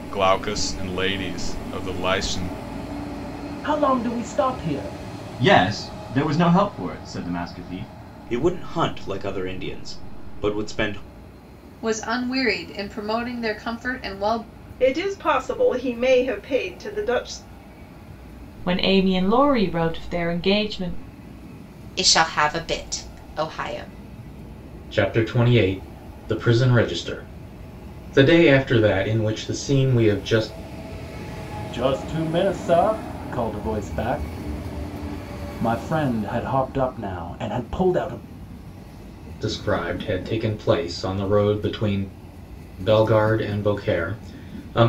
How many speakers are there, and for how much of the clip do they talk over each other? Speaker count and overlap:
9, no overlap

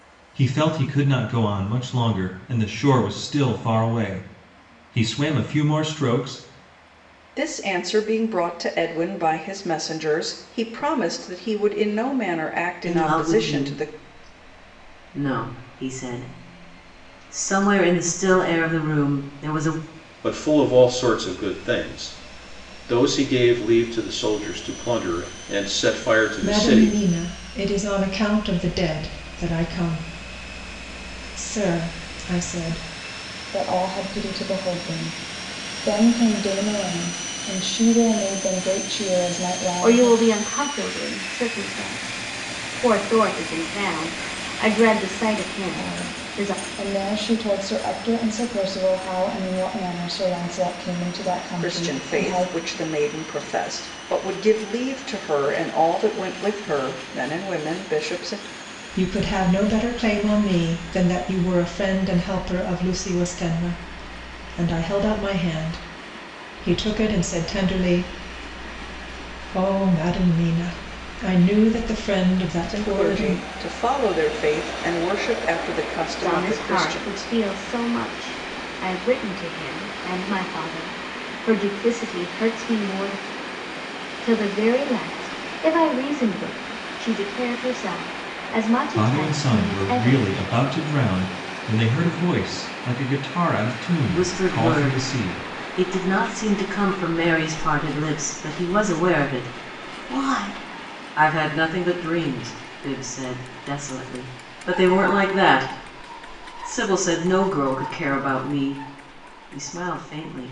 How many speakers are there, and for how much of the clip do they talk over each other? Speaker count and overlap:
7, about 8%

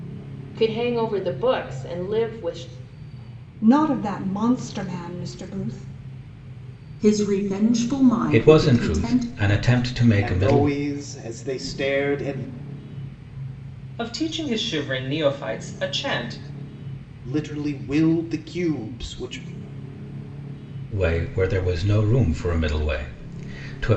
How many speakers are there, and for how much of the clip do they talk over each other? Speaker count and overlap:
6, about 7%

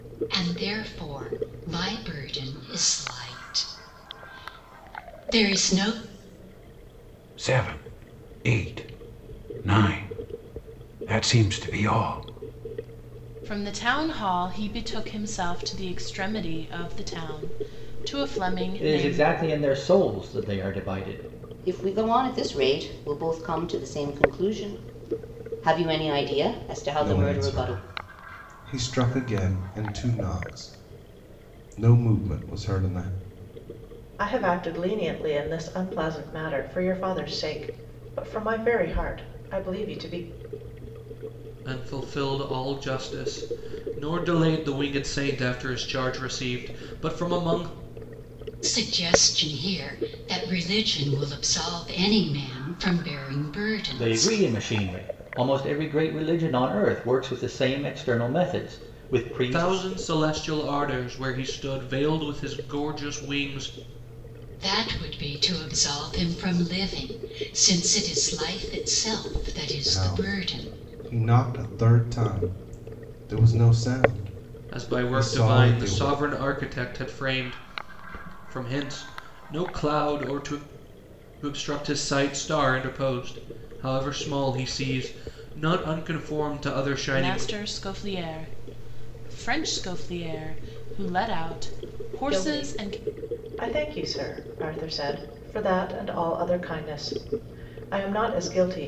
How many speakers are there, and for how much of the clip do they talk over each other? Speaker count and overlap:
8, about 5%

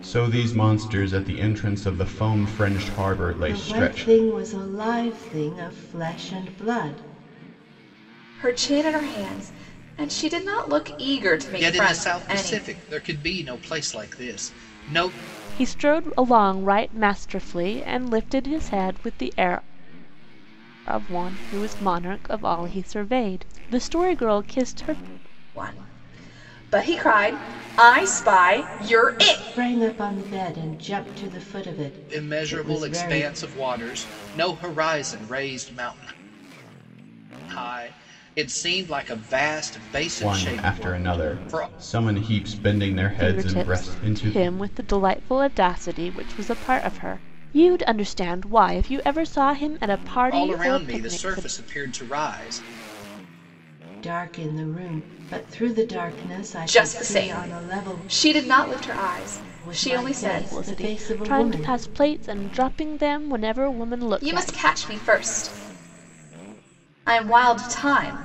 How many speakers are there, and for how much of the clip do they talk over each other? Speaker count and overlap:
5, about 17%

